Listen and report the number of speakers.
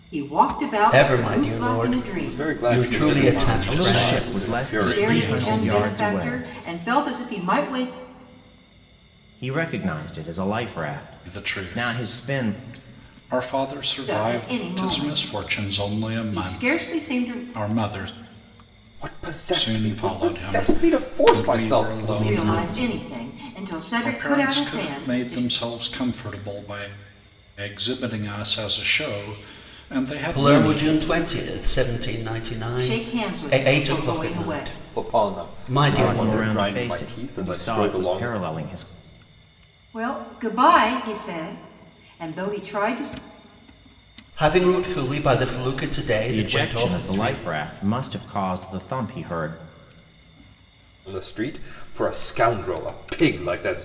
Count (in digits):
5